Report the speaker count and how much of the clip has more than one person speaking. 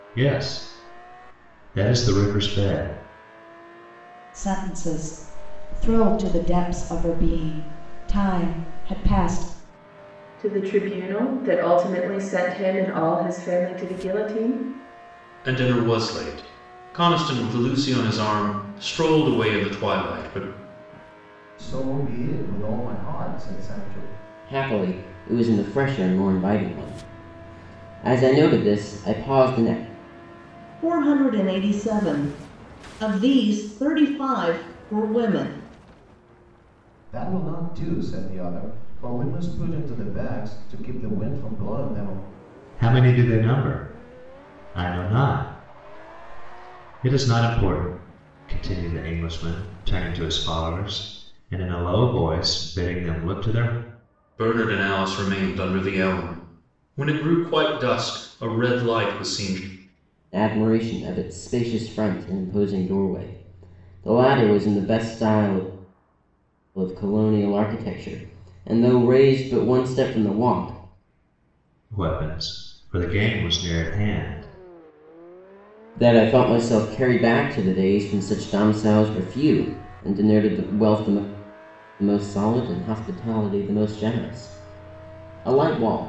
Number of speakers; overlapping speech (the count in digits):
7, no overlap